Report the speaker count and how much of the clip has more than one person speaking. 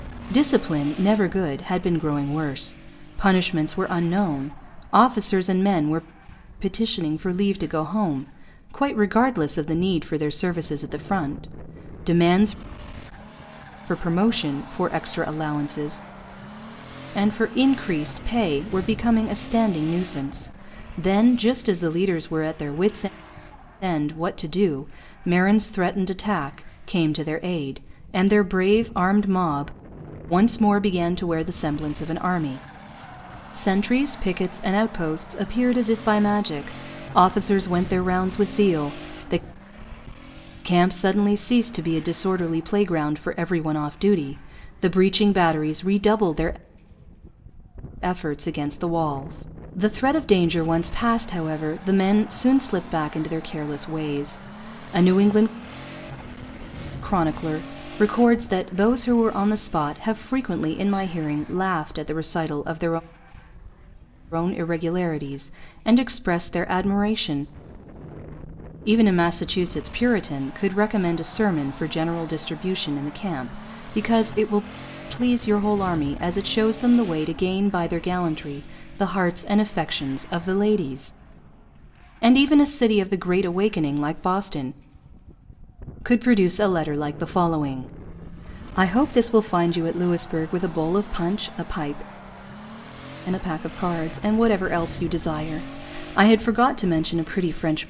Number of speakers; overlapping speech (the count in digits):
1, no overlap